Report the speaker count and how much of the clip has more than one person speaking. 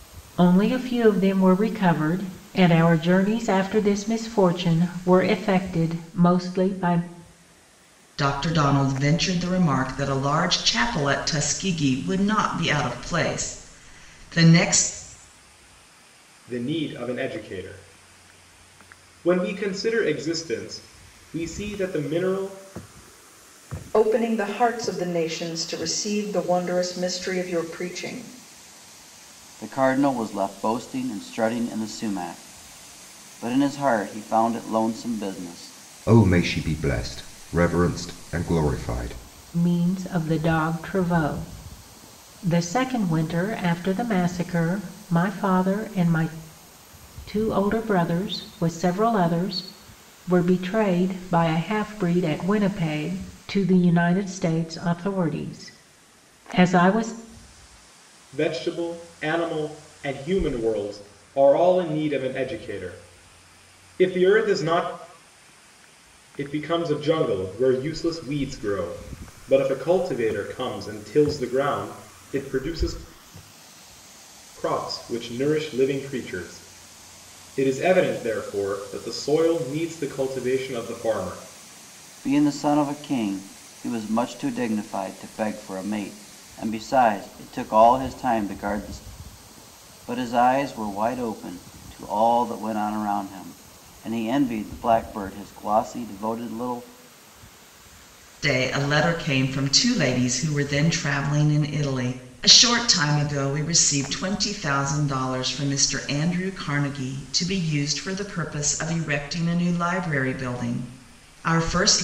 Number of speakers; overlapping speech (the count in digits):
6, no overlap